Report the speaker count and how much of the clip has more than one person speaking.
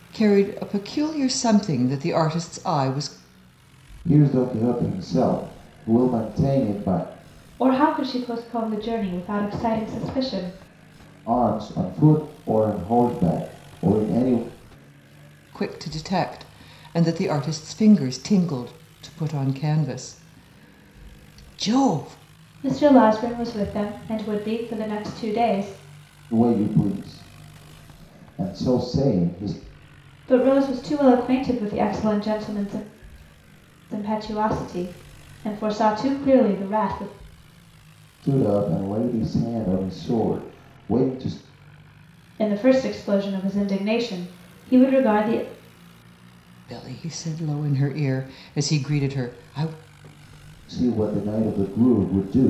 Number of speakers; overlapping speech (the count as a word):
three, no overlap